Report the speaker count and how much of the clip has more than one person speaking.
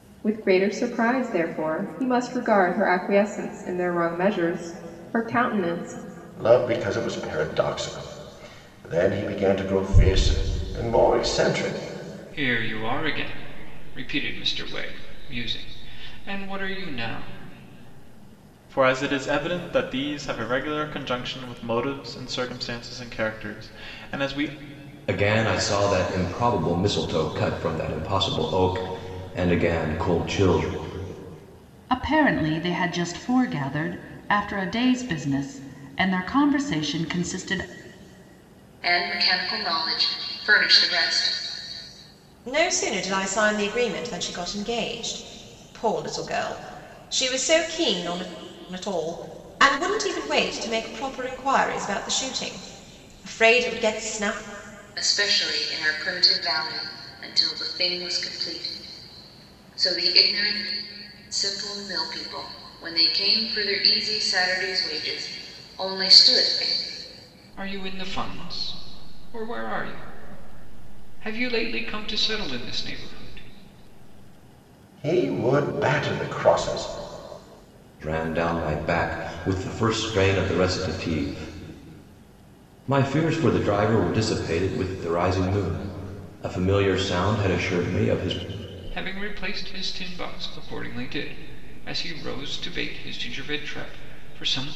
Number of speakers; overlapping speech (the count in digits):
8, no overlap